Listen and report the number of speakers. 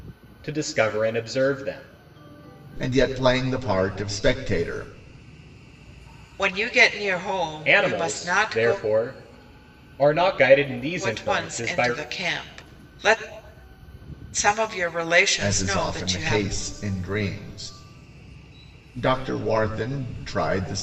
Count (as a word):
three